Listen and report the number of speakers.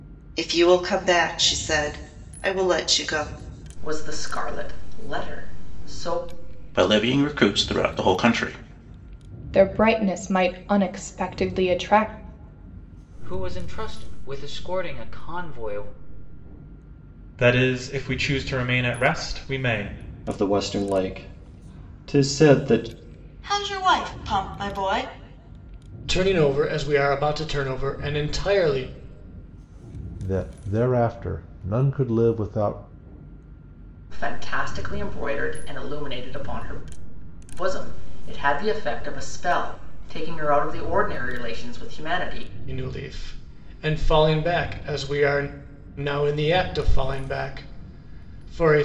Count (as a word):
ten